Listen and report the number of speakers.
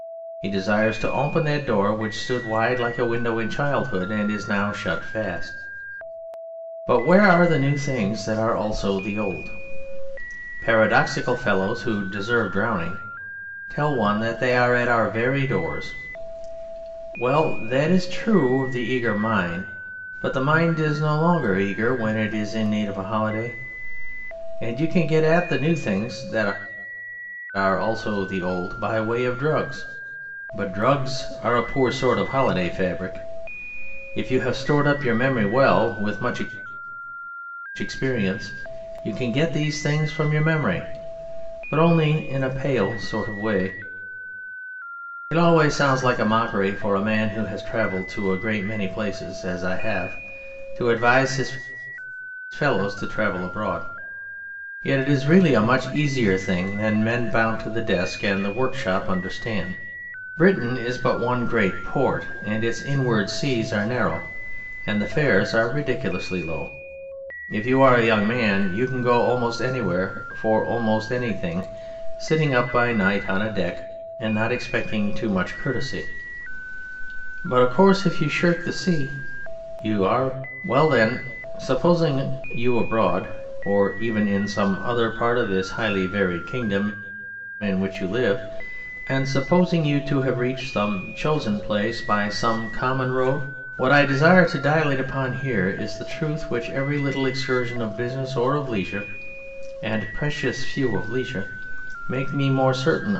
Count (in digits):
1